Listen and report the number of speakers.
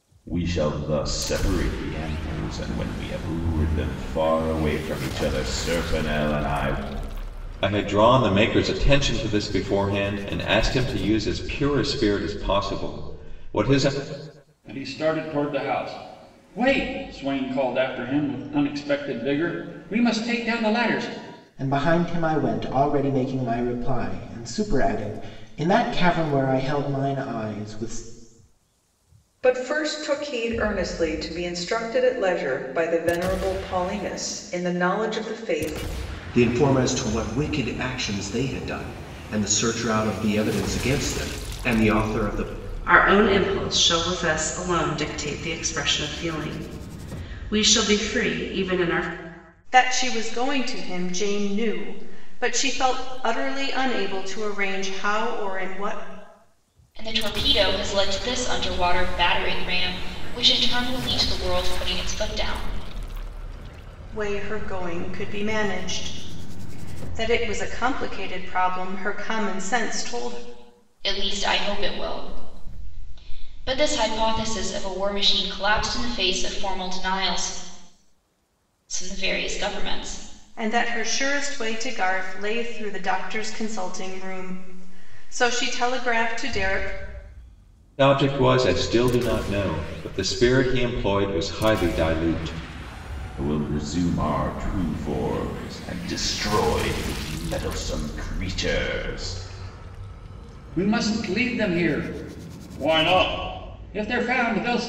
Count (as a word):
nine